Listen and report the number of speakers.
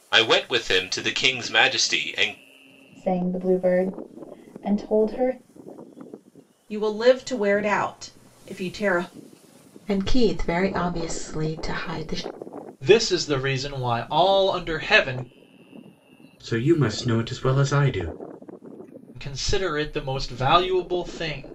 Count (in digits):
6